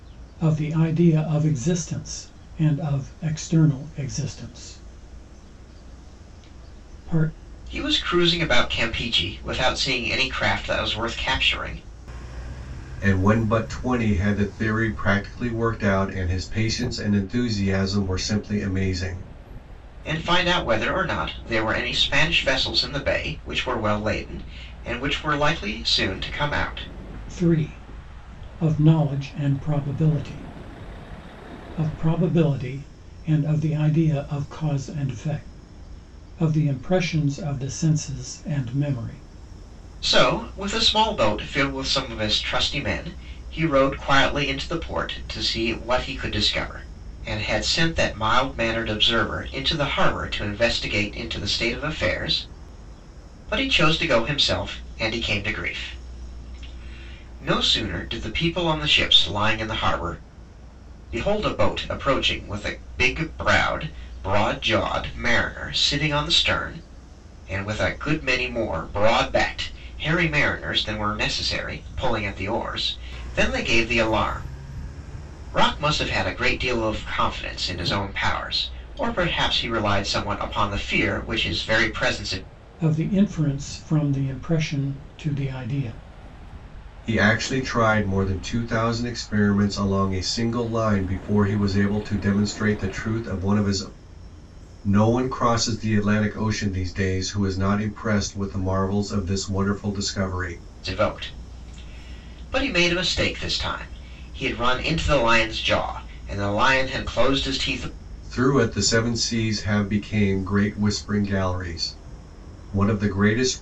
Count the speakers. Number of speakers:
3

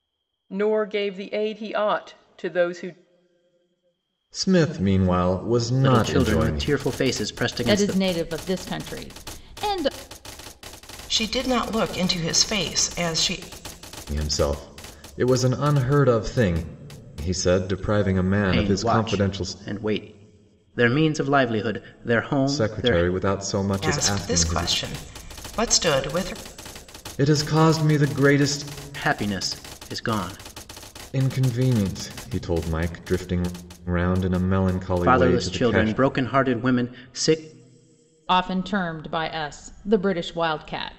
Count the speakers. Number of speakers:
5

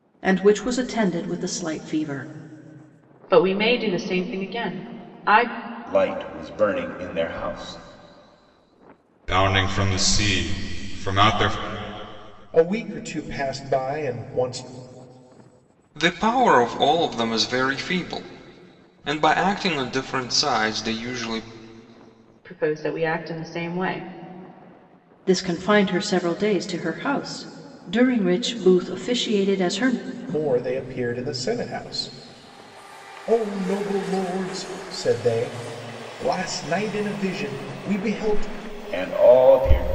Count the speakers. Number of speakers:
6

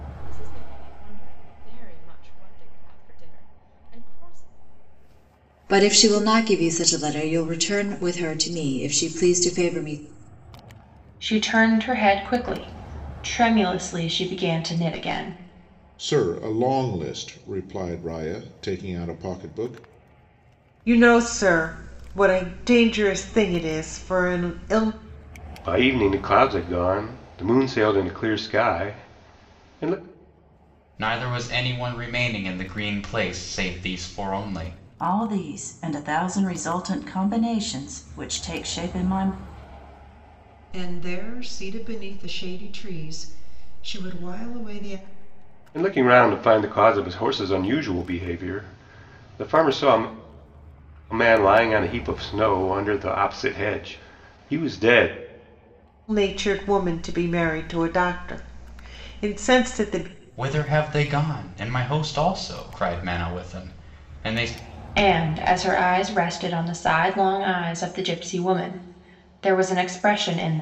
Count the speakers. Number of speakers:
9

